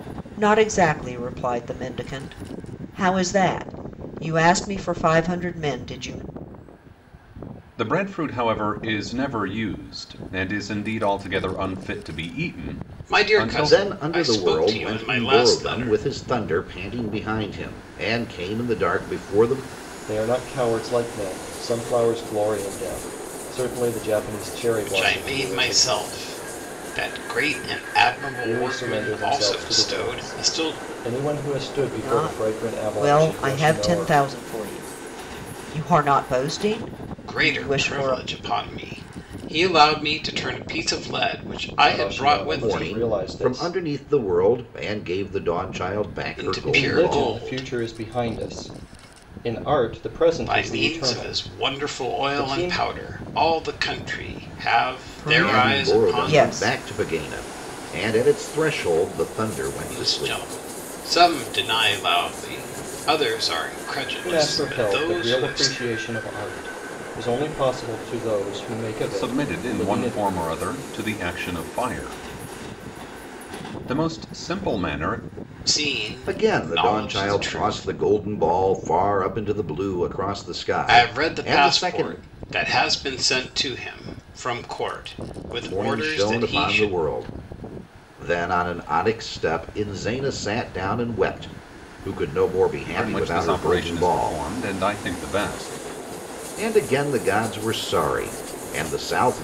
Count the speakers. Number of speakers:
5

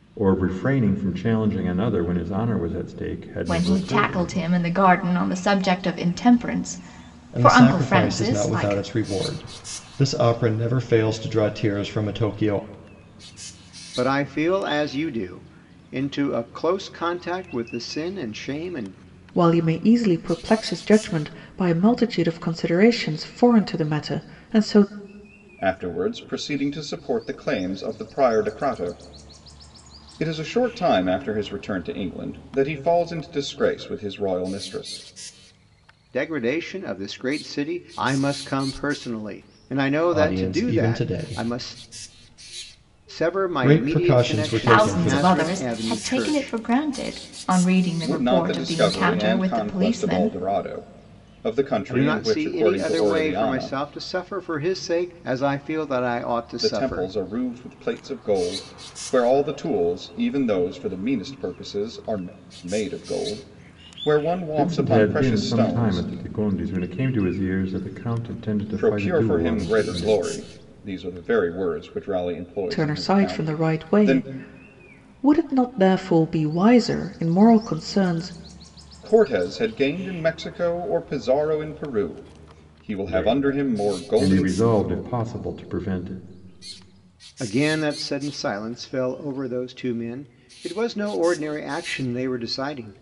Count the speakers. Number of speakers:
6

